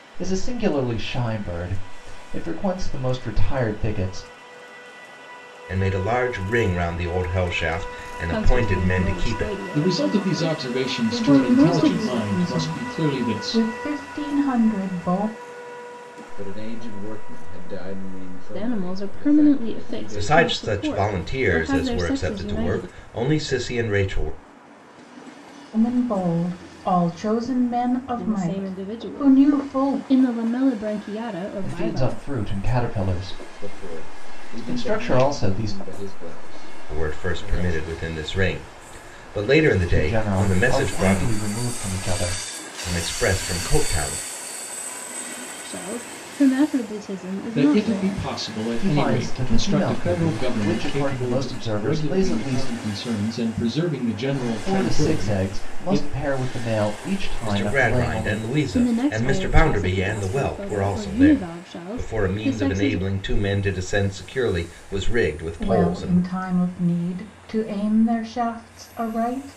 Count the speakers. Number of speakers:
6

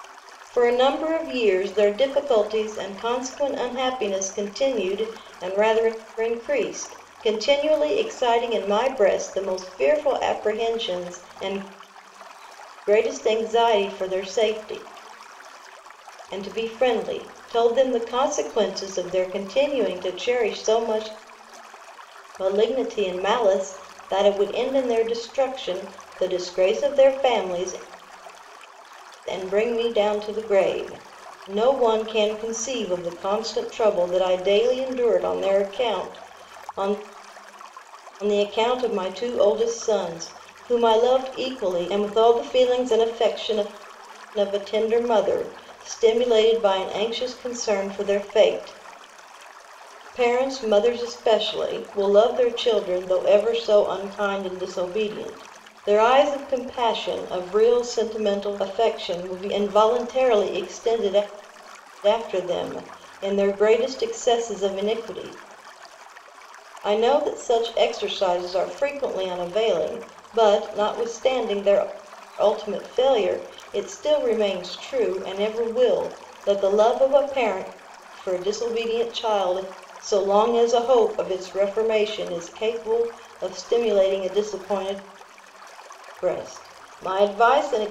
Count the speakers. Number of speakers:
1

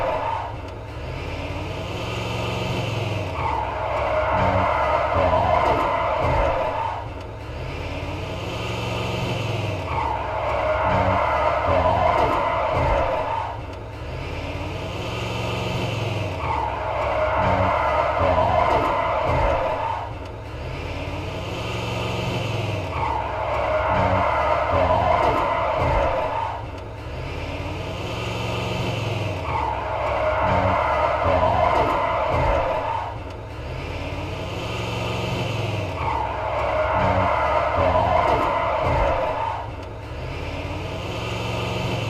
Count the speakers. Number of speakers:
0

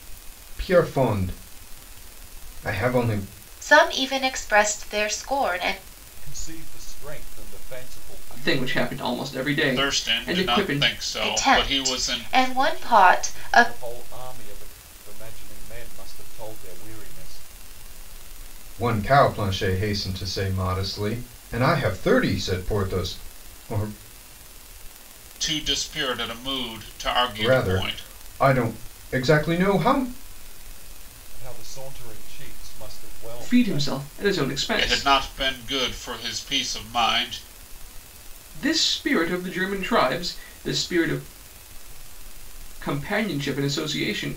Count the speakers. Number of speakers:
5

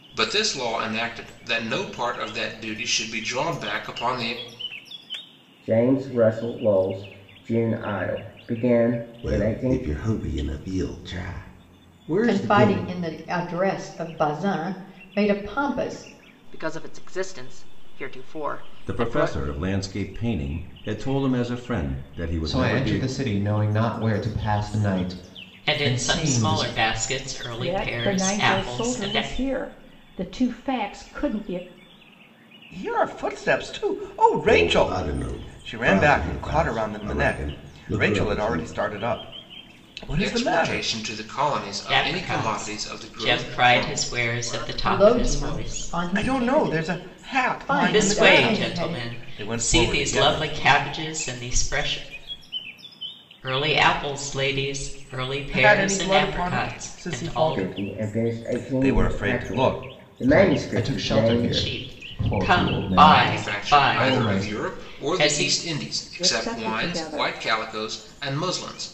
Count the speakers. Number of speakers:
10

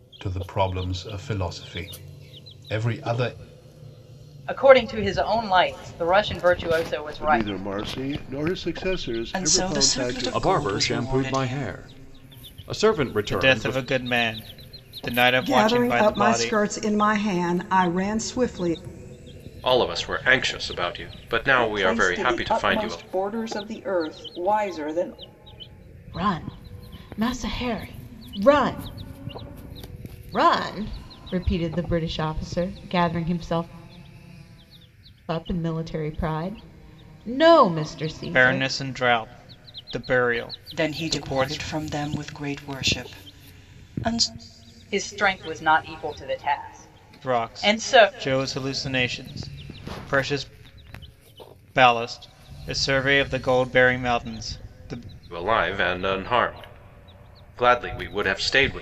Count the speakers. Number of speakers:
10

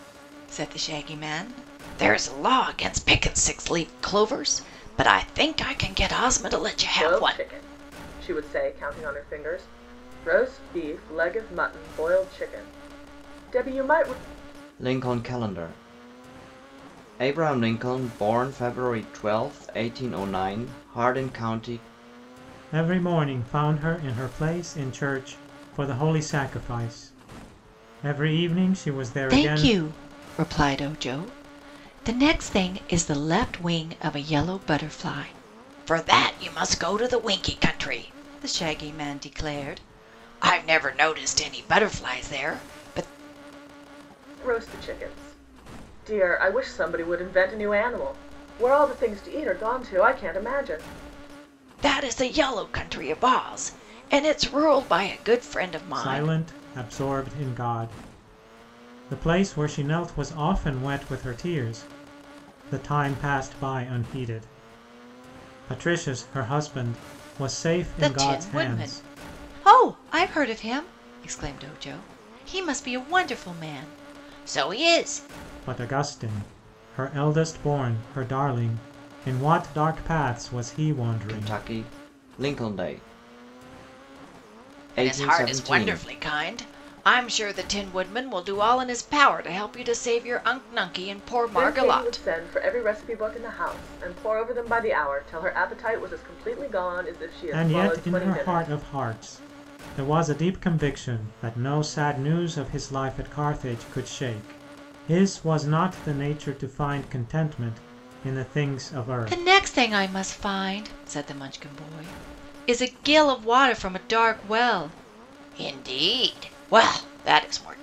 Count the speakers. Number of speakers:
4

